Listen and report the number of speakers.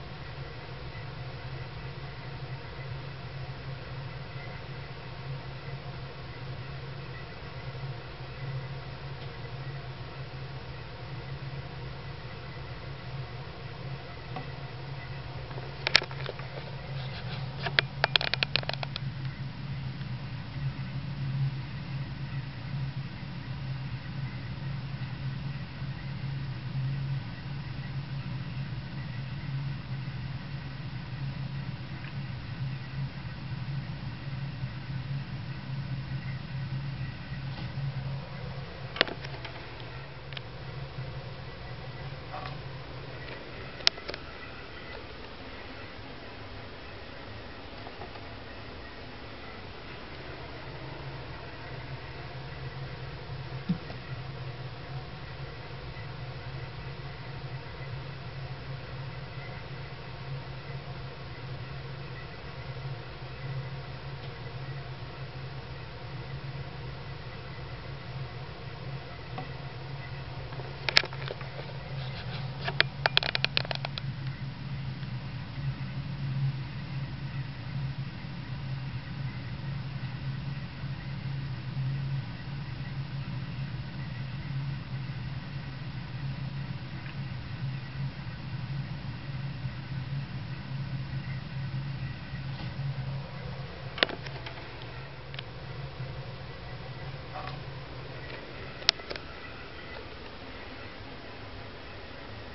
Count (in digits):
0